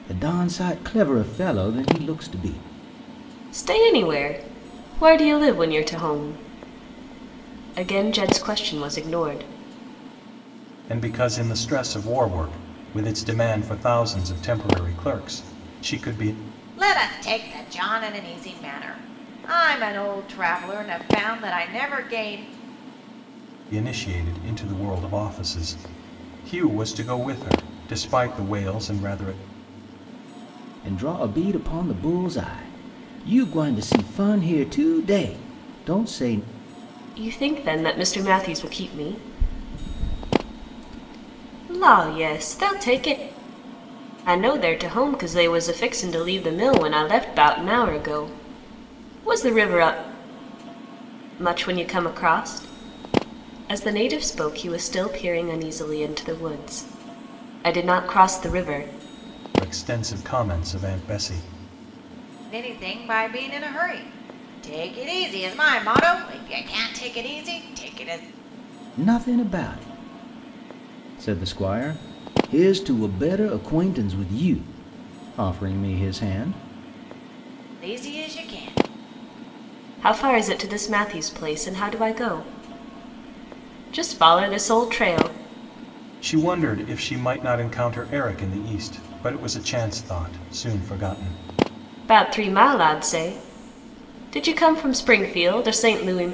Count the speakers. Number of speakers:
four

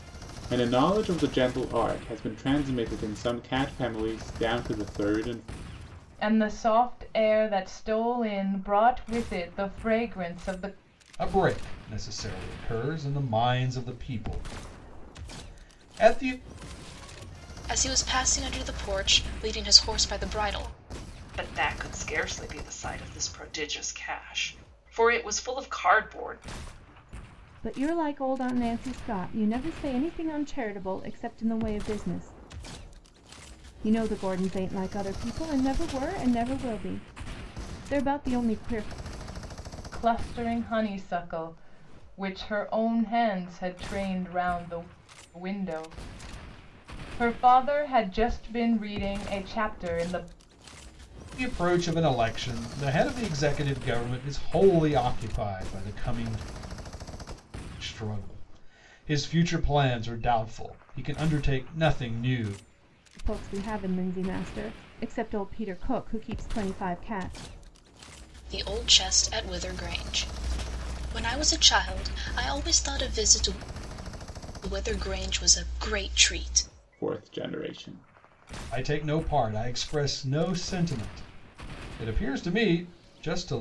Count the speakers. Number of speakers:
six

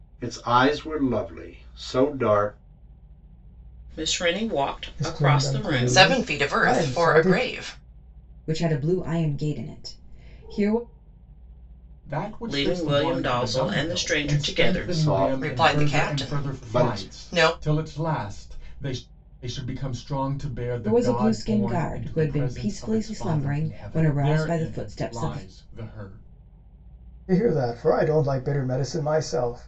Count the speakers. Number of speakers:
six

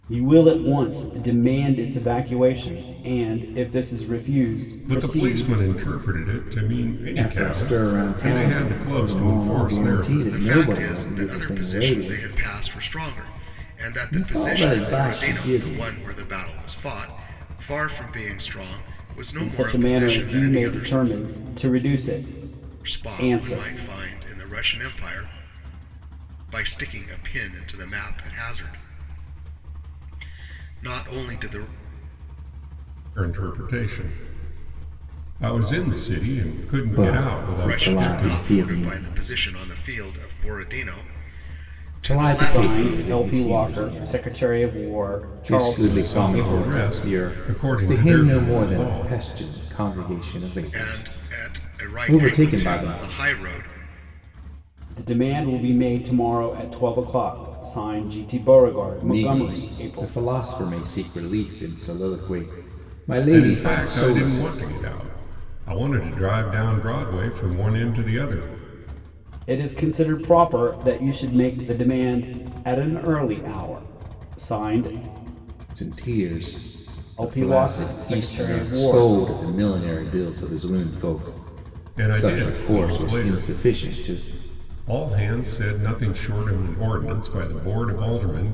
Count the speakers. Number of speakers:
four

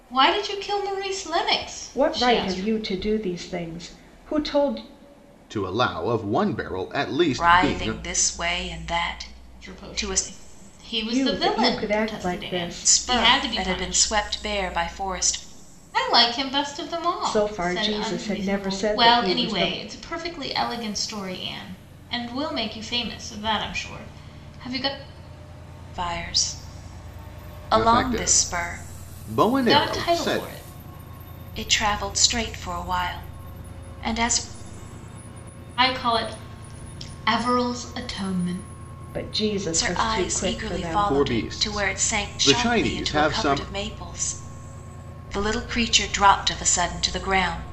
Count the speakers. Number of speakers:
four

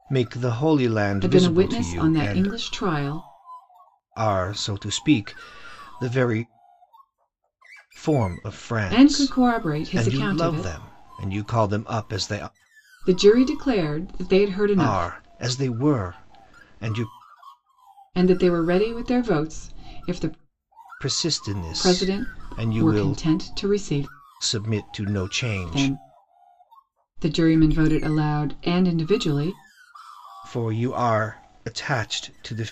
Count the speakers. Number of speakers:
two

